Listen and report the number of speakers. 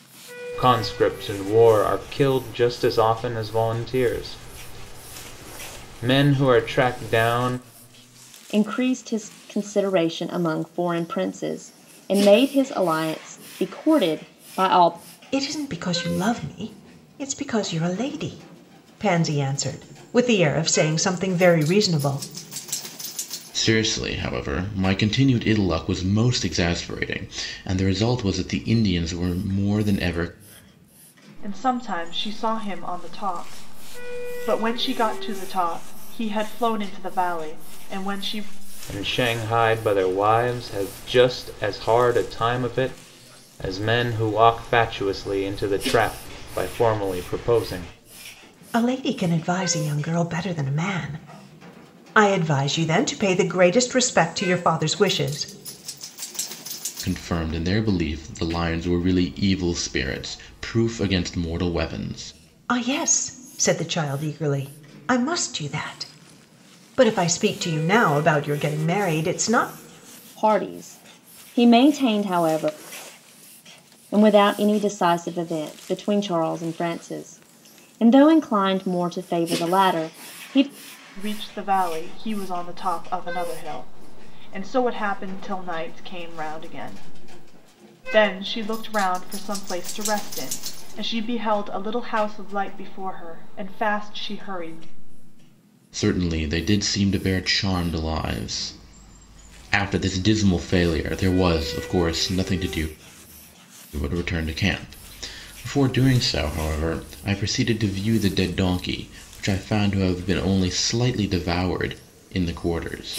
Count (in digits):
5